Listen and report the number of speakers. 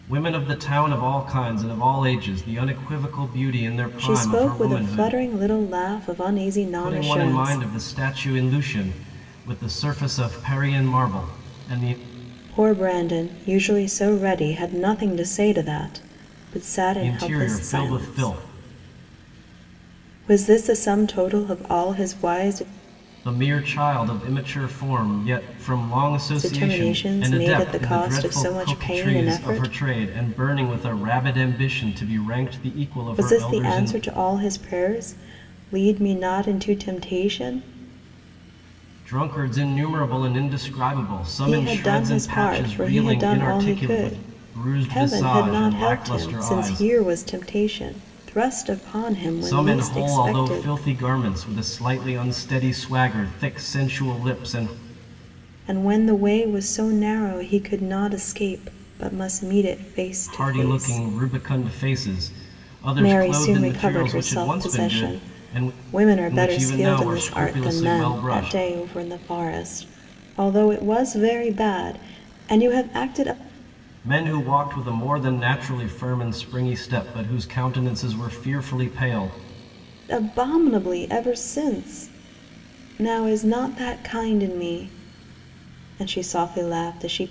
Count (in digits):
2